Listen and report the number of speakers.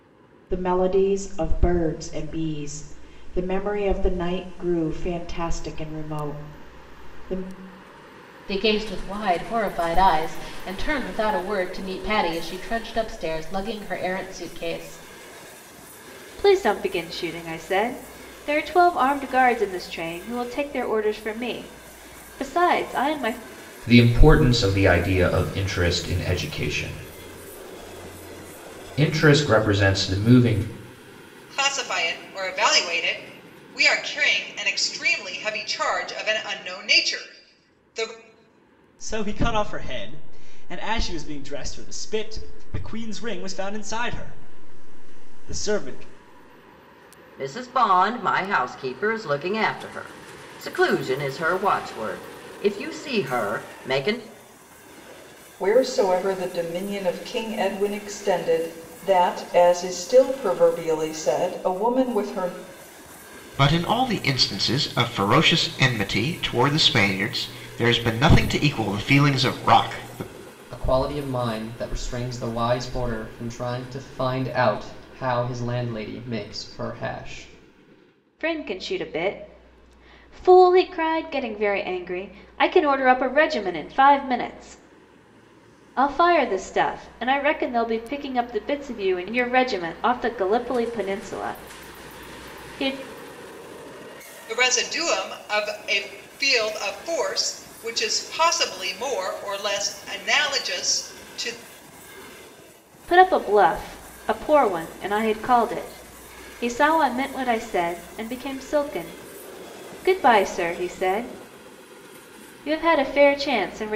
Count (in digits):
10